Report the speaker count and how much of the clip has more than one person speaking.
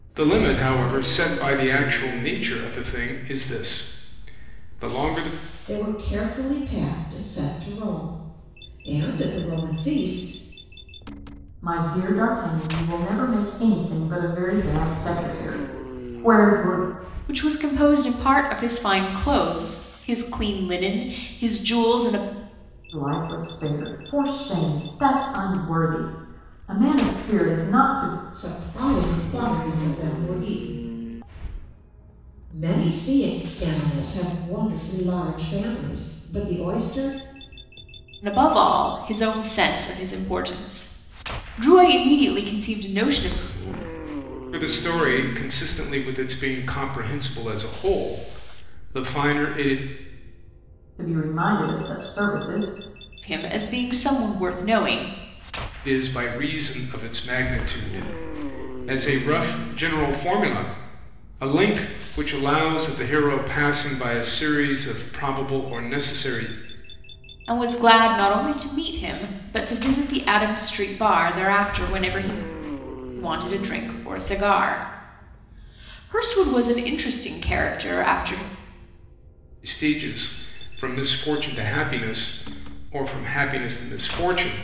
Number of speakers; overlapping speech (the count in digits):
4, no overlap